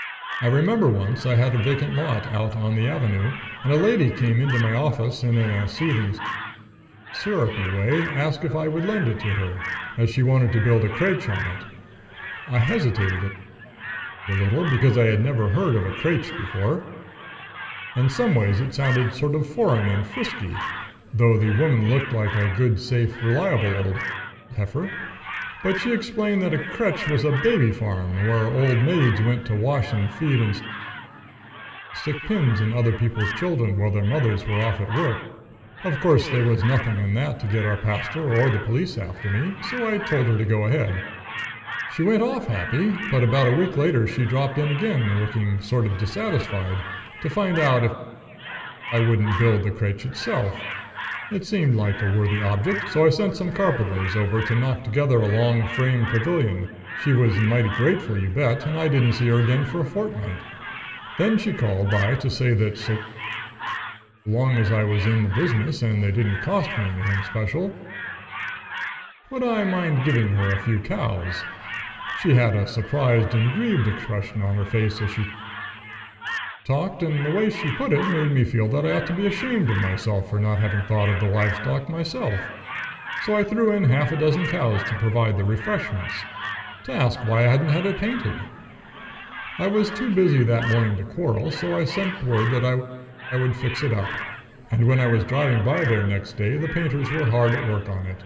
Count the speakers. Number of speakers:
one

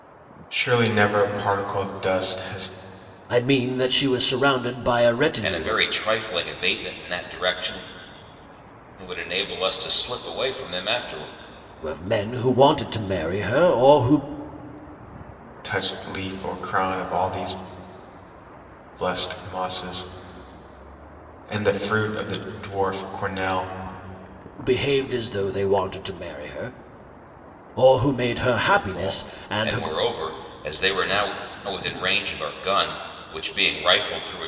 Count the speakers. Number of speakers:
three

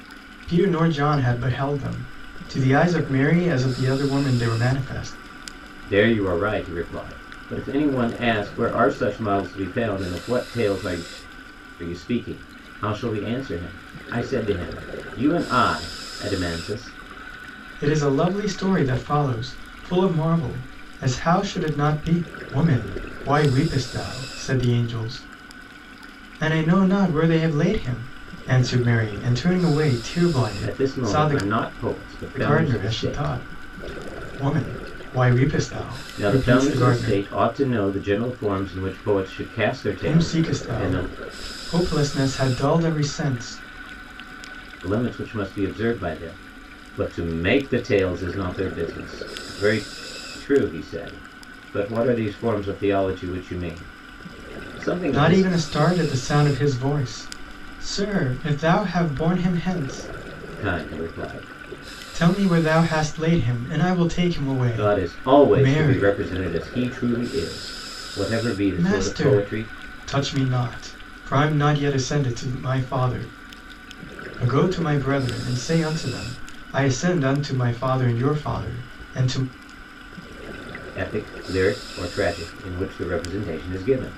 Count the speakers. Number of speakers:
two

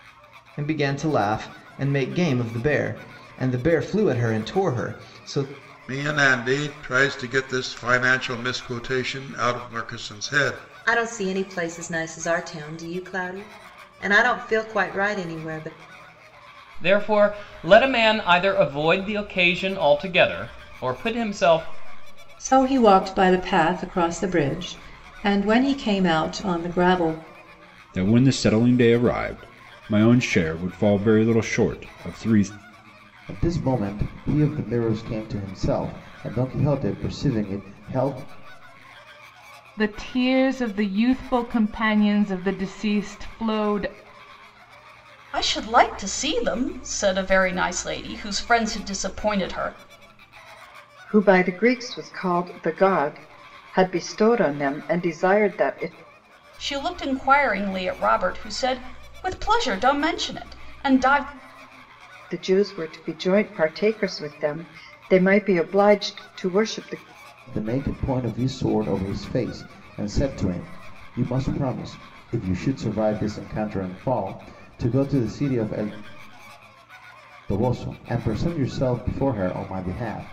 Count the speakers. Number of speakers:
ten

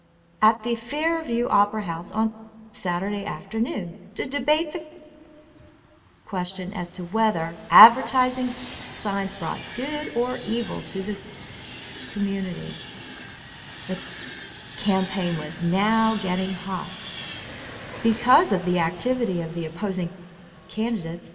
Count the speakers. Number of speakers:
one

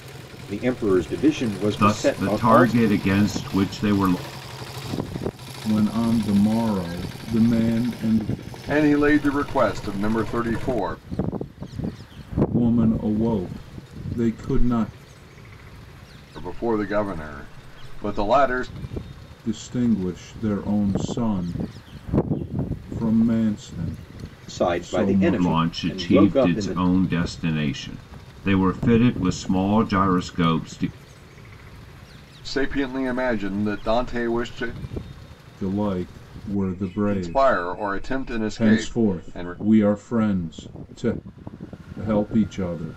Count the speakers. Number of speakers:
four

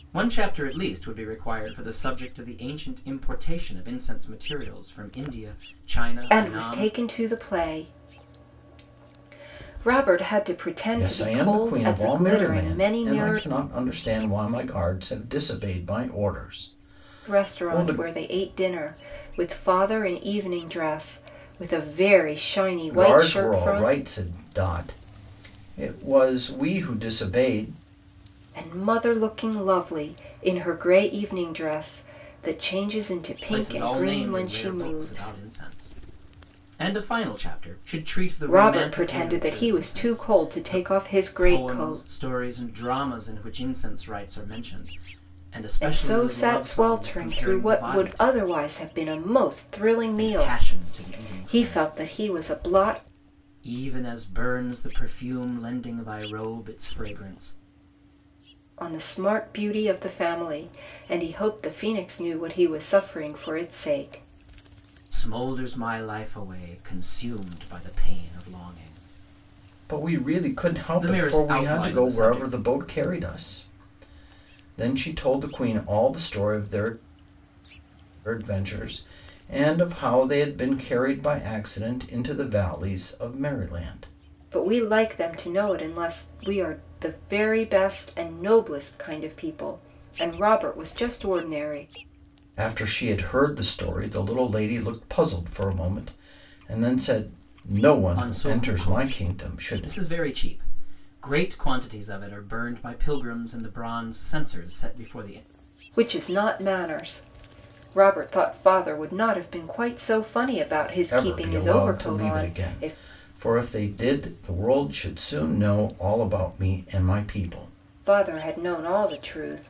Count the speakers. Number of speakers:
three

